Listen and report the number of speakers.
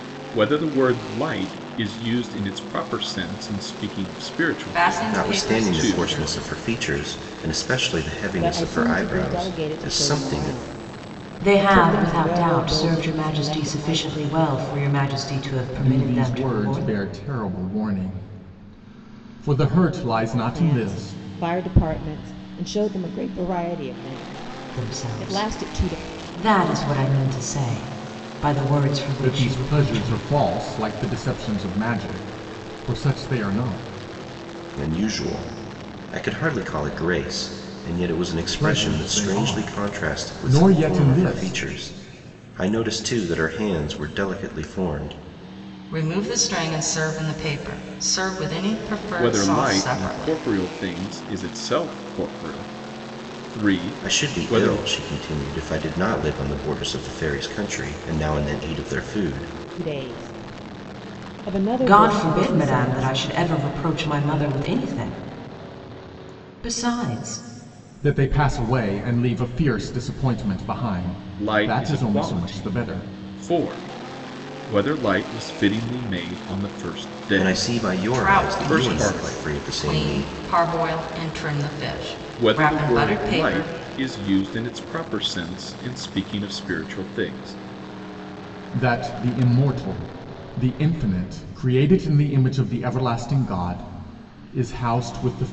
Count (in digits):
6